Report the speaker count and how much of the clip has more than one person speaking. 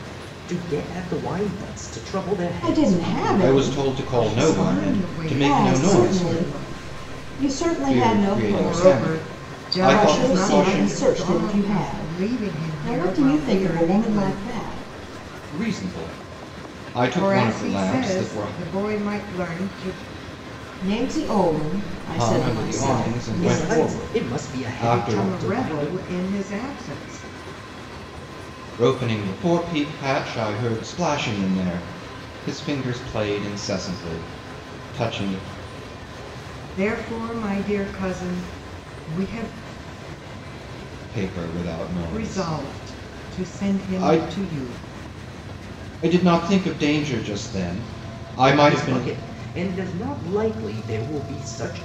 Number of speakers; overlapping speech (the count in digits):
4, about 36%